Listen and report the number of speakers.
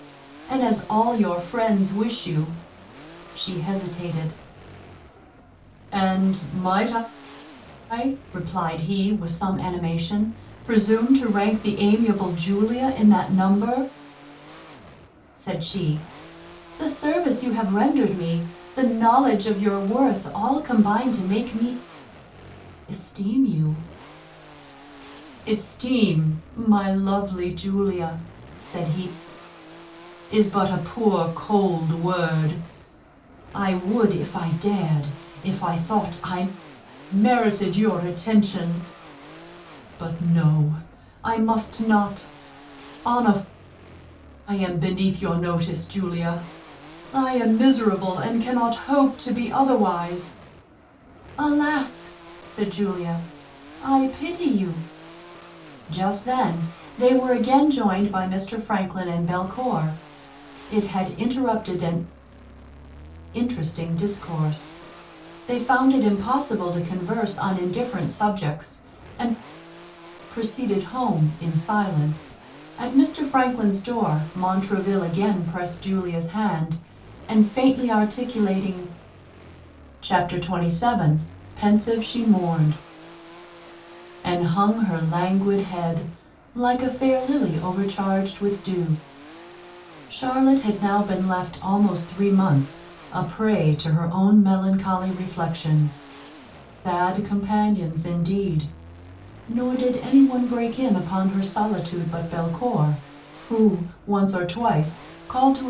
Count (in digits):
1